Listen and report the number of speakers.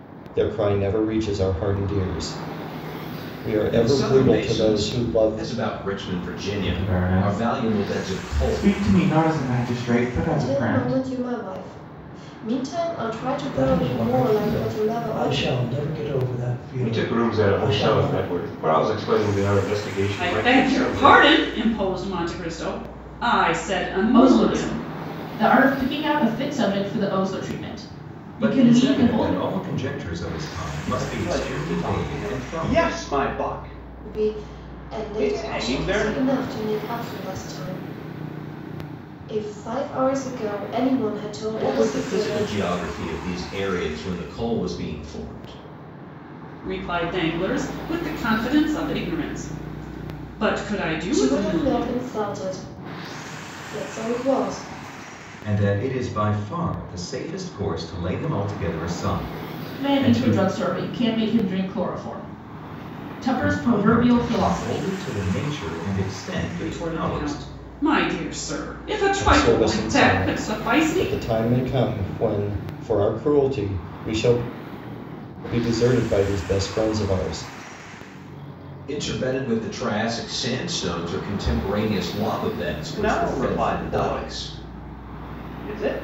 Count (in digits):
10